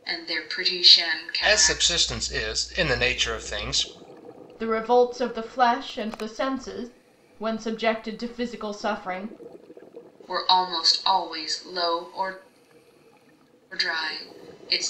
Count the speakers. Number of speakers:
three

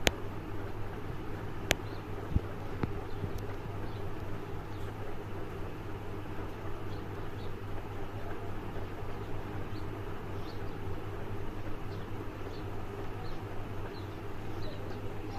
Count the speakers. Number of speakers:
zero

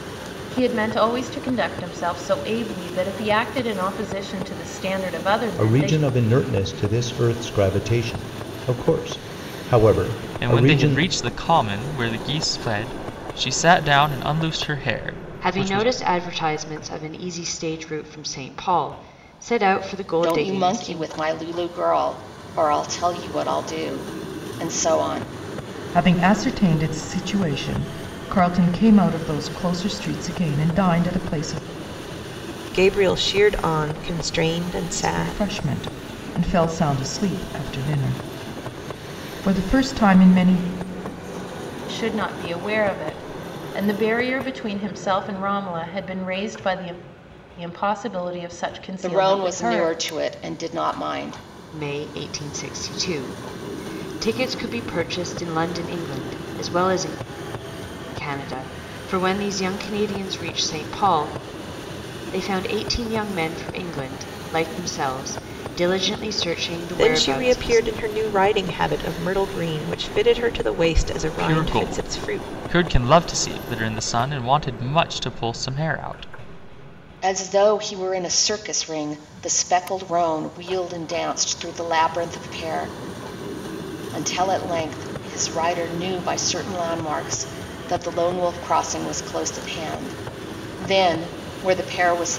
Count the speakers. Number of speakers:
seven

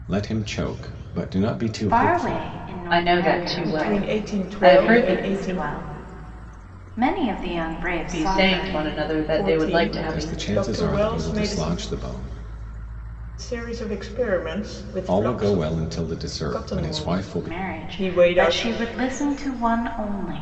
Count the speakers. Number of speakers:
four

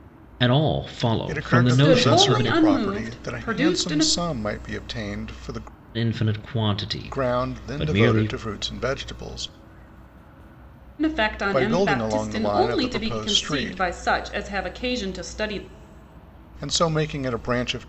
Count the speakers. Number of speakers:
three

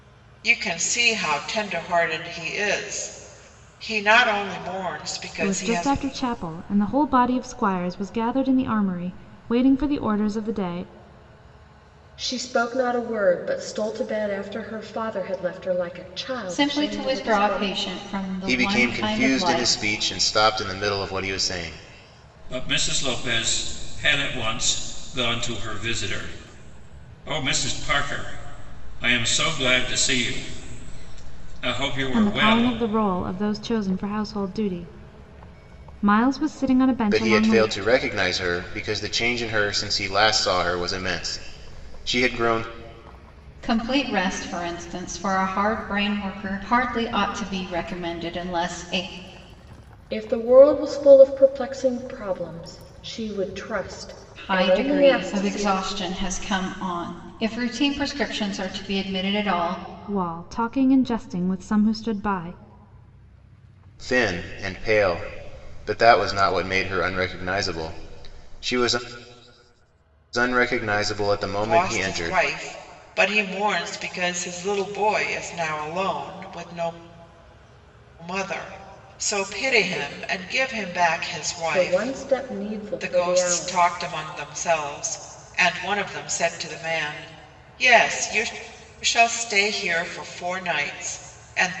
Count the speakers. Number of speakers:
six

